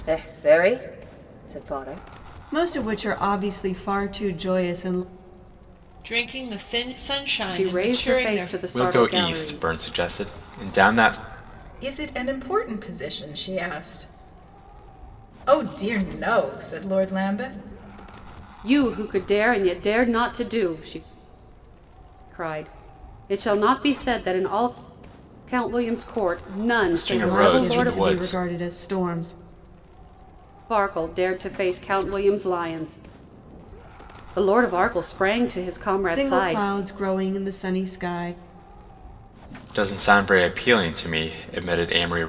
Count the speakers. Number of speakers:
six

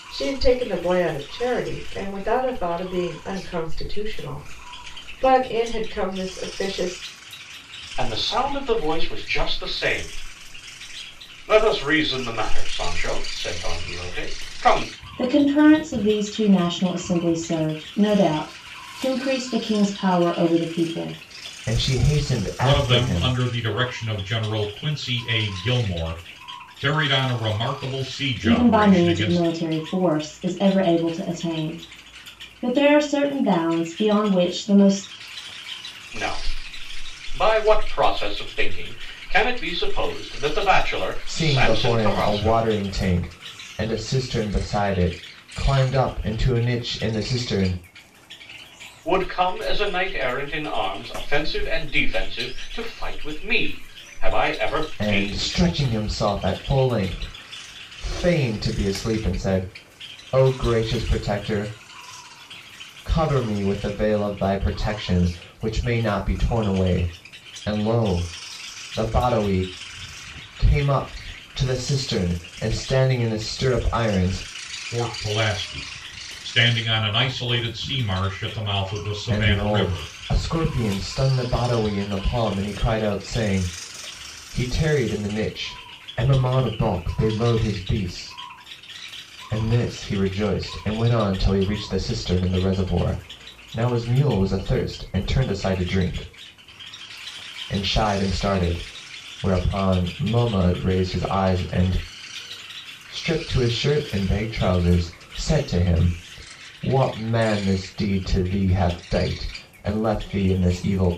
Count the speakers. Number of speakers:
five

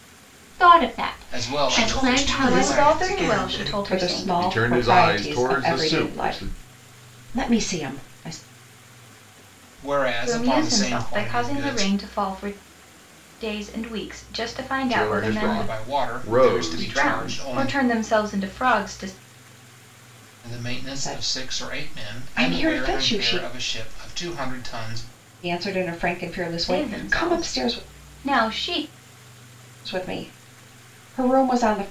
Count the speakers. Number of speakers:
six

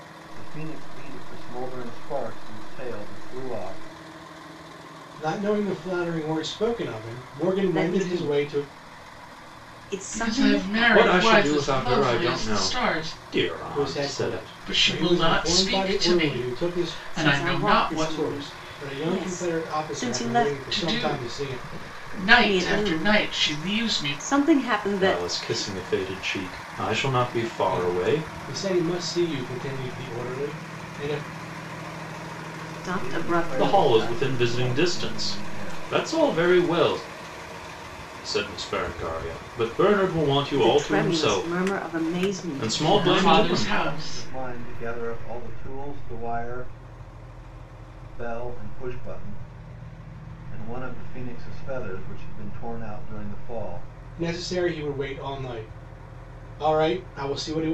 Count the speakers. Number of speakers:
five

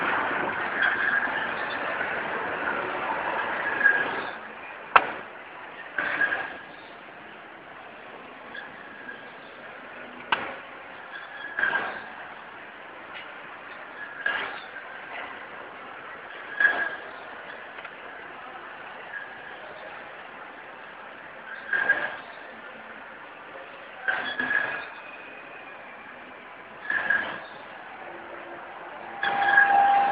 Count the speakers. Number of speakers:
zero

